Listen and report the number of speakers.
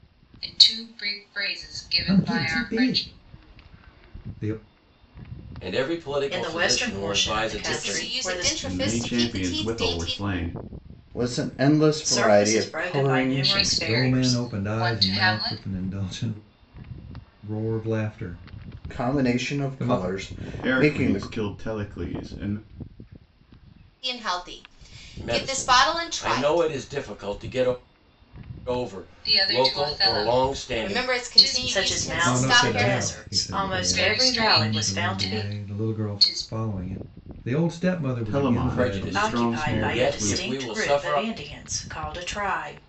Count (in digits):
7